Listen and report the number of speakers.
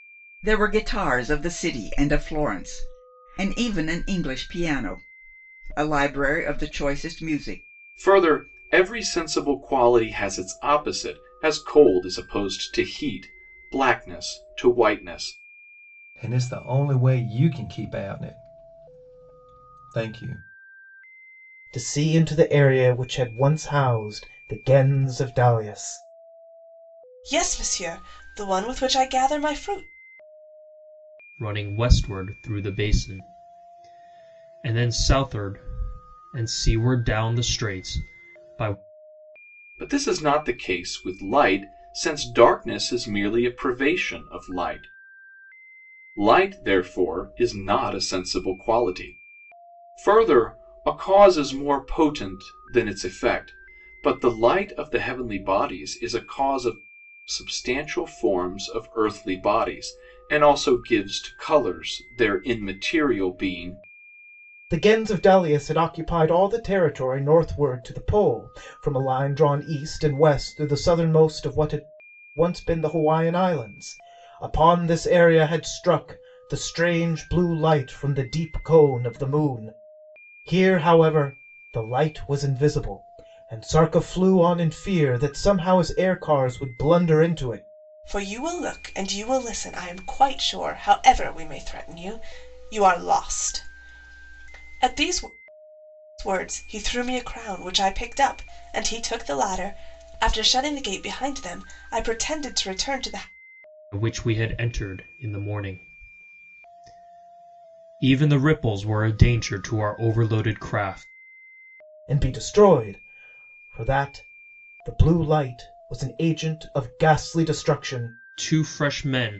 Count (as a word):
six